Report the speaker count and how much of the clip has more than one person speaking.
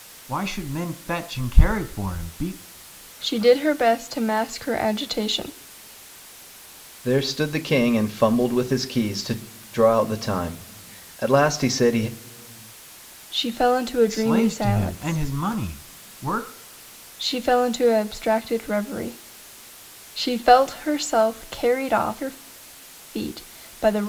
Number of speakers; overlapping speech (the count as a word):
three, about 5%